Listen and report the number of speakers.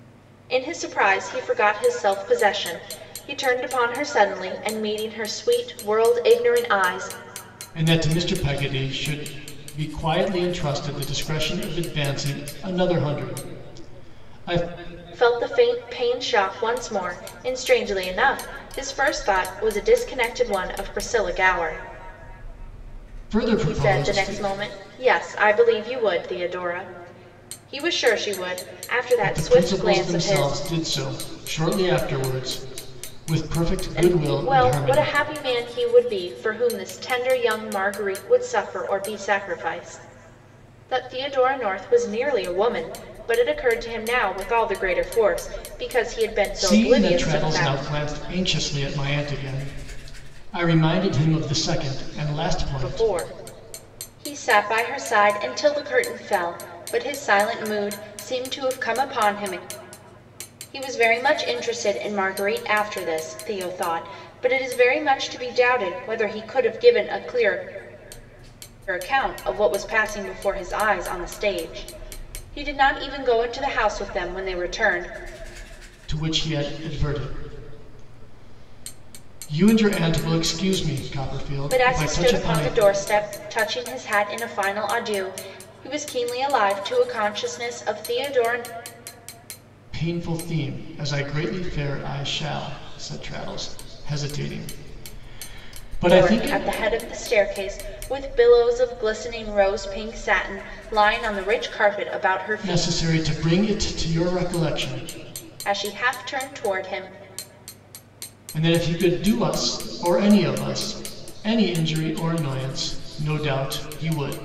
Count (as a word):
two